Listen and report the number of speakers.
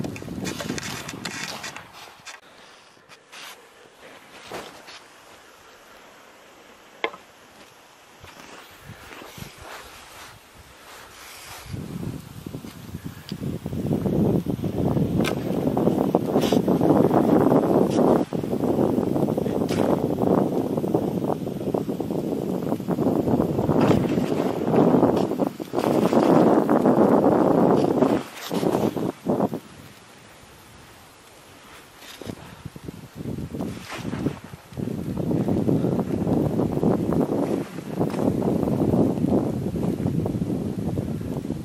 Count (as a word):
zero